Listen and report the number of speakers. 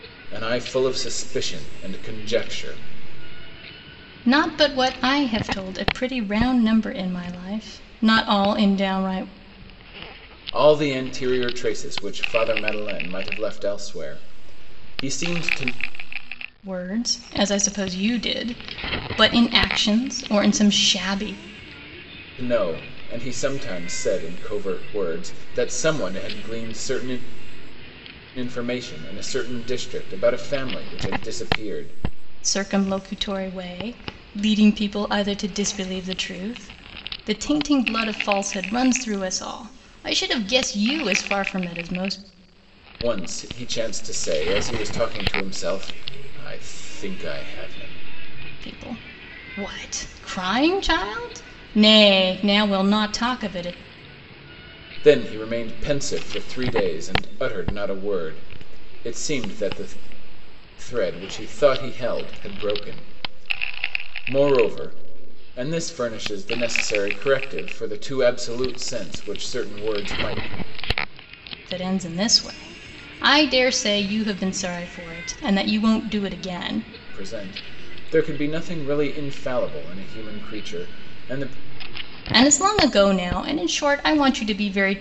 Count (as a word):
two